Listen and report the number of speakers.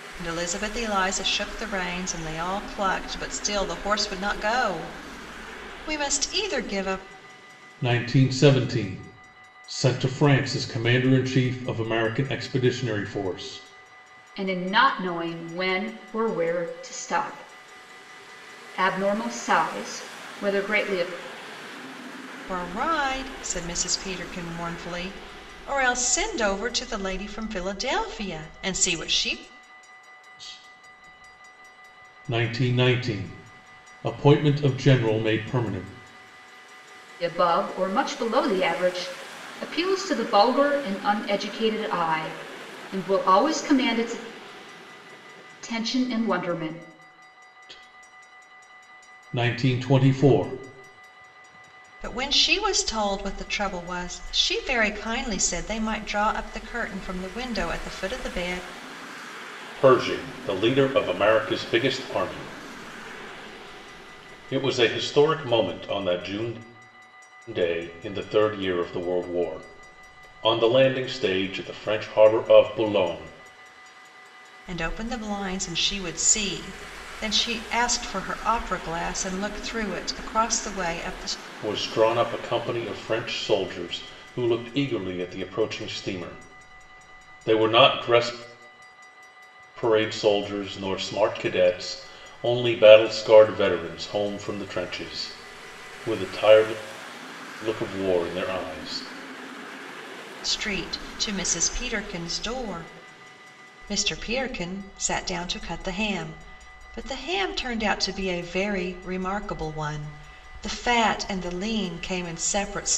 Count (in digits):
3